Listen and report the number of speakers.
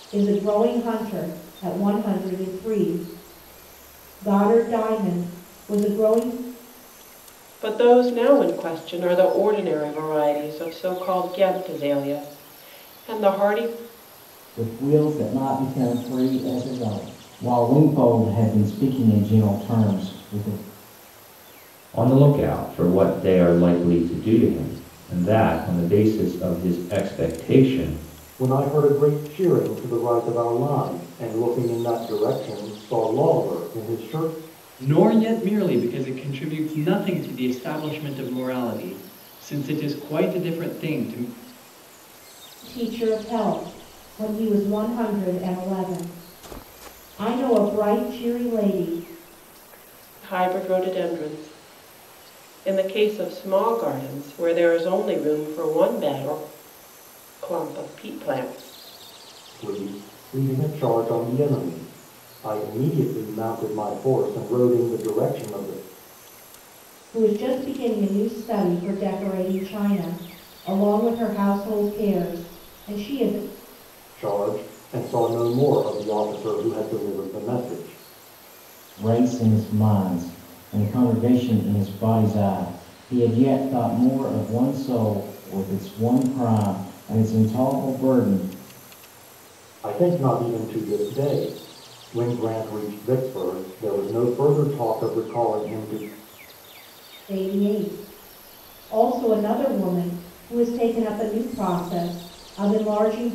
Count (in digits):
6